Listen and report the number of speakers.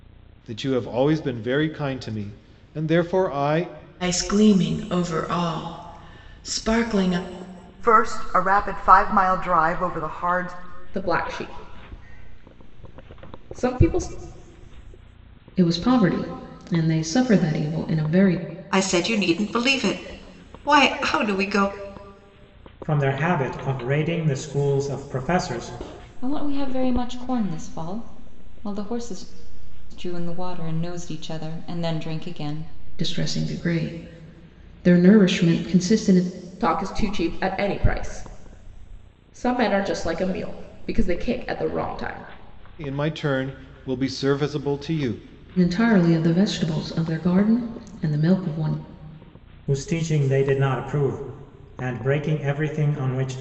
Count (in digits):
8